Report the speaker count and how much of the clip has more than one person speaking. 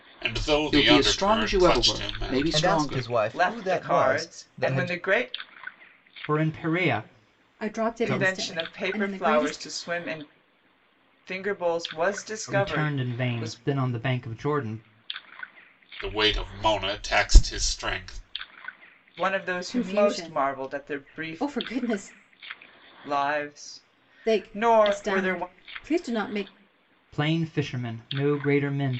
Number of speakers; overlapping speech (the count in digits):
6, about 36%